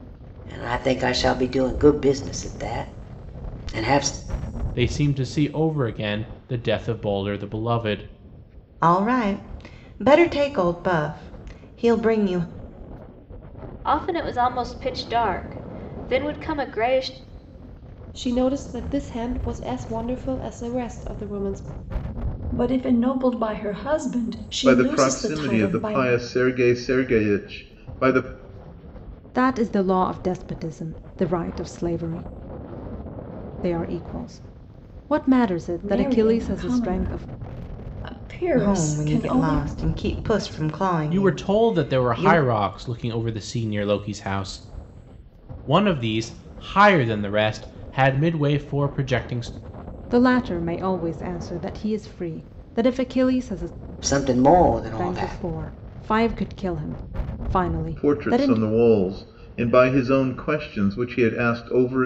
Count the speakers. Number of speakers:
8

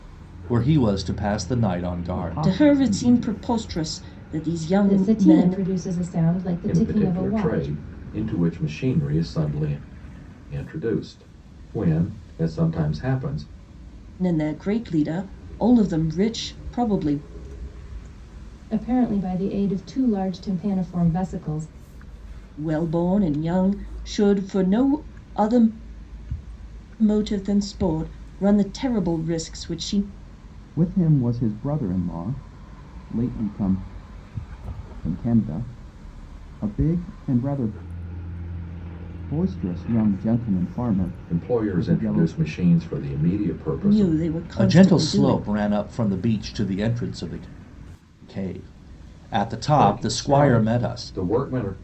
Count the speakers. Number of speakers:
5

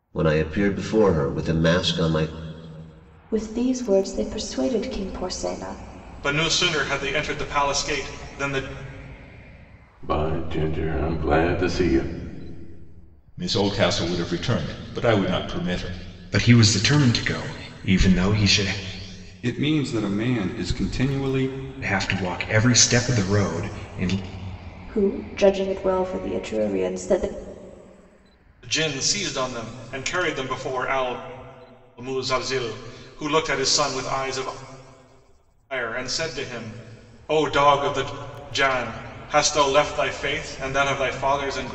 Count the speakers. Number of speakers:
7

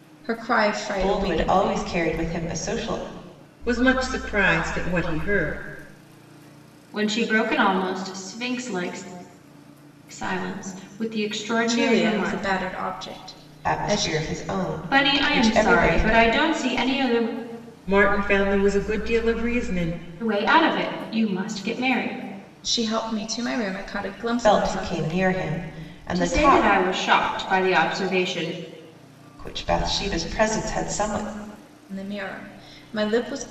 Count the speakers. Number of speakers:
4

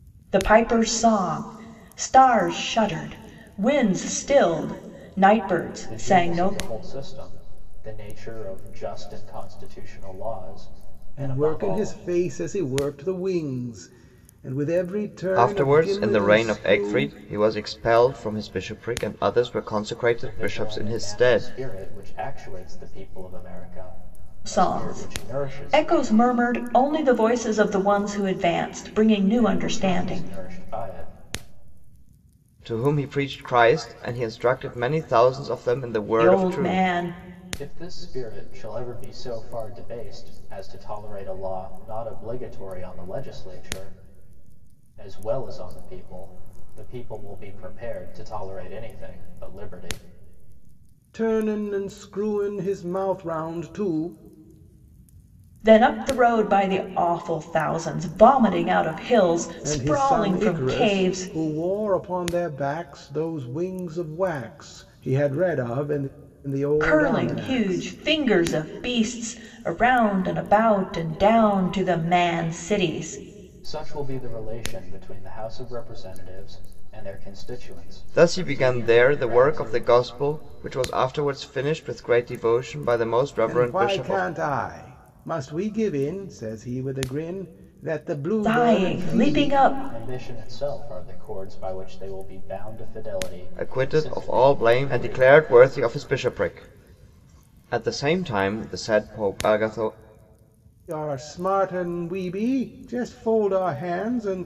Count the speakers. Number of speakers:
4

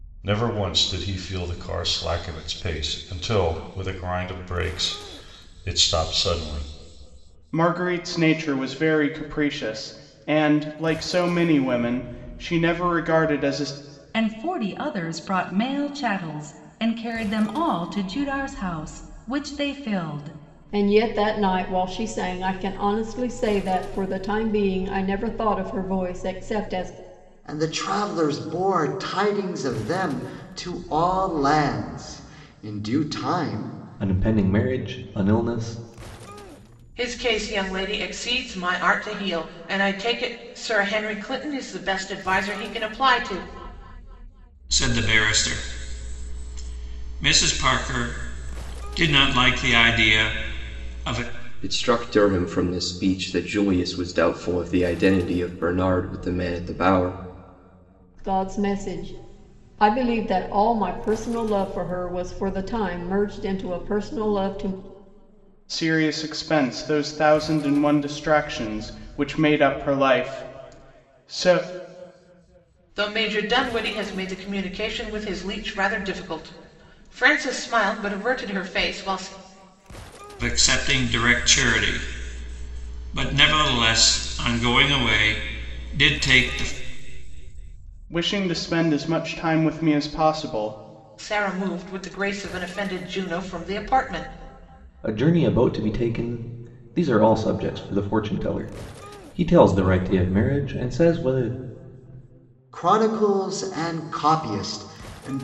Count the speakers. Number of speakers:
9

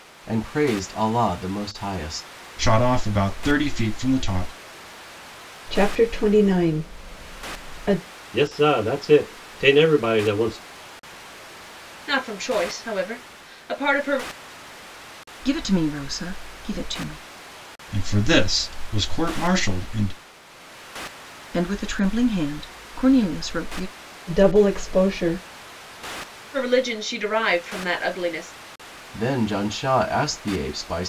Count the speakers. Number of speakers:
6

